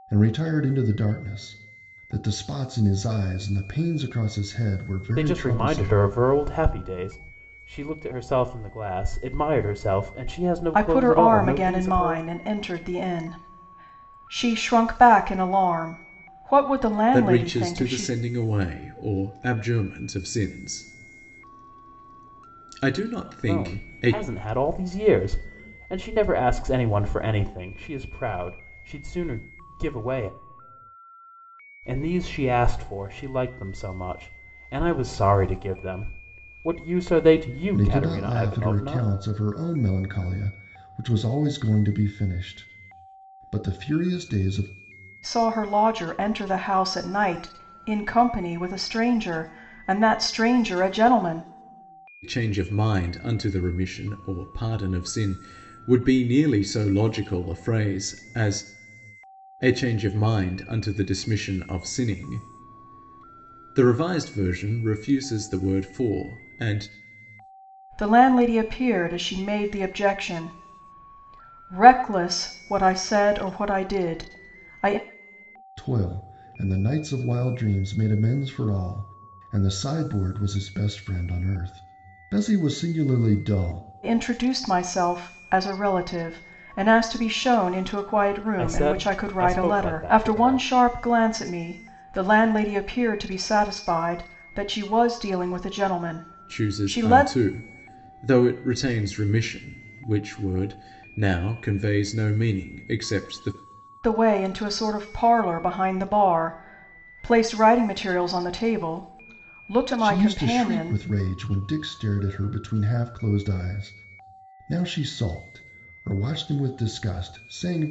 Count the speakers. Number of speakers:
four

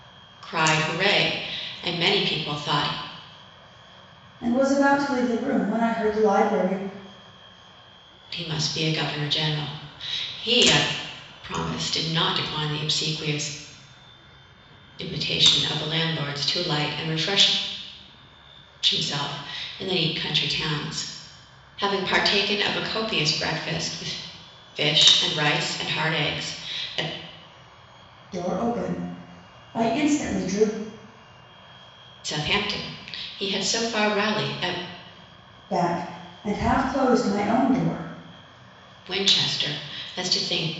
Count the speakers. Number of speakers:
two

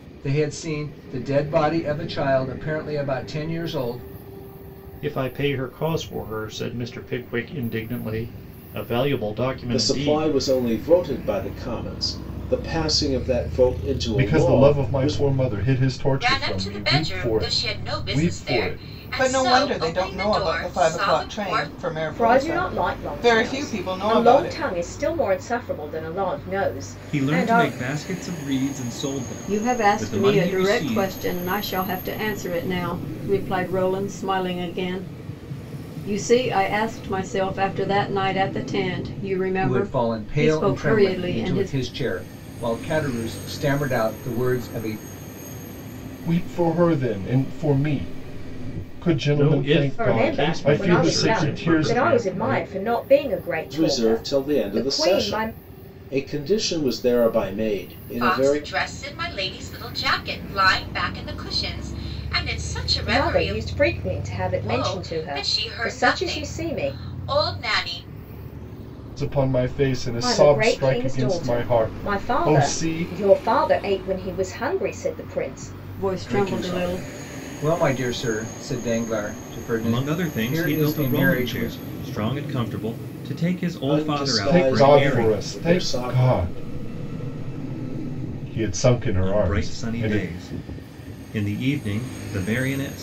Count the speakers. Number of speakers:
nine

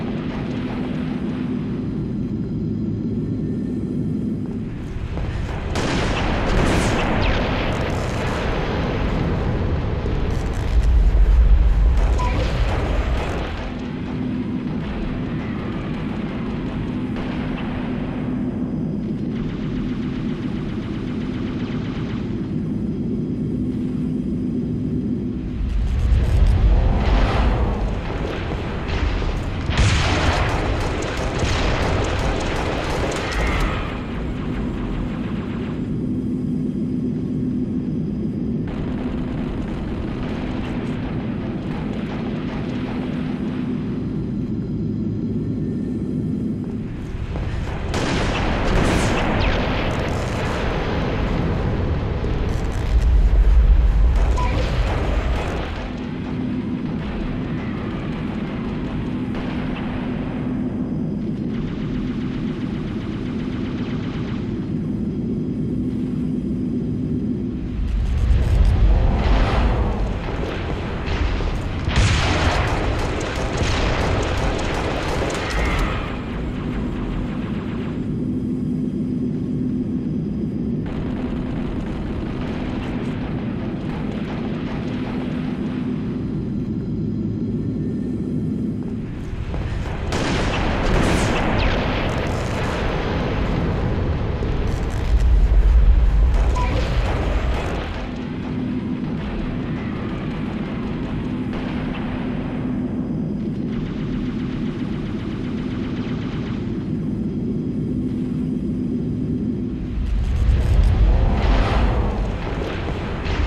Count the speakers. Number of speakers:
zero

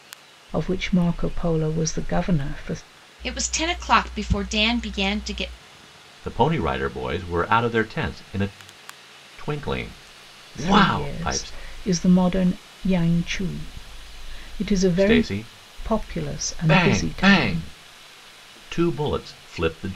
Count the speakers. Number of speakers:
three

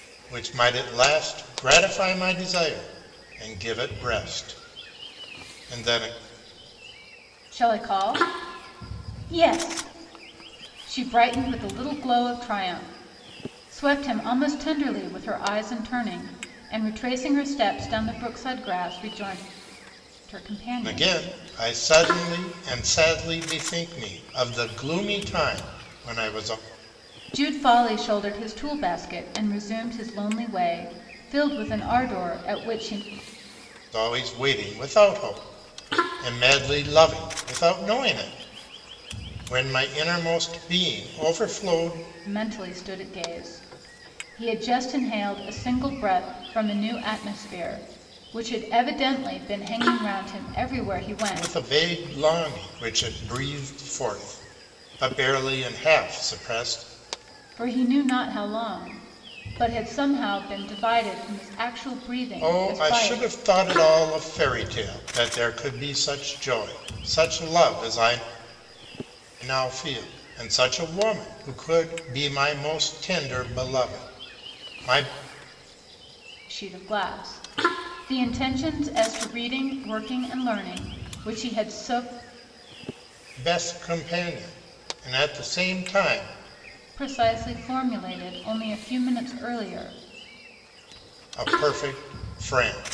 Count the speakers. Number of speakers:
two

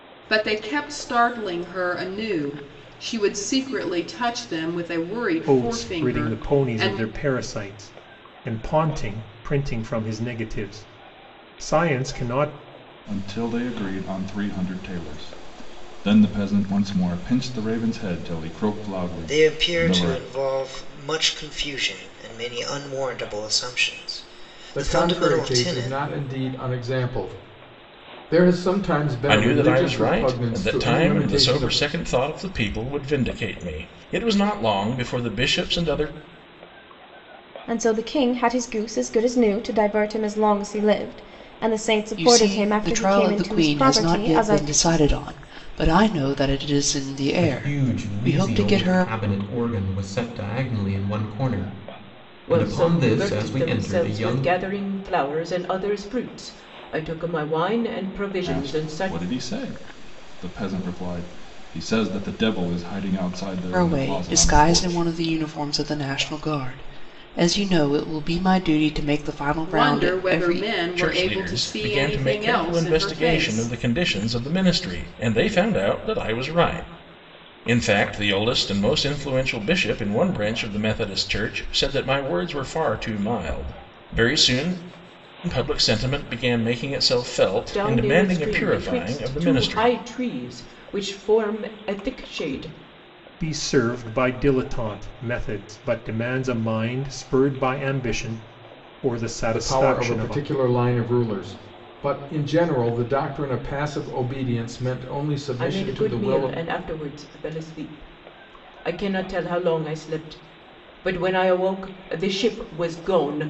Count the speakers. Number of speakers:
ten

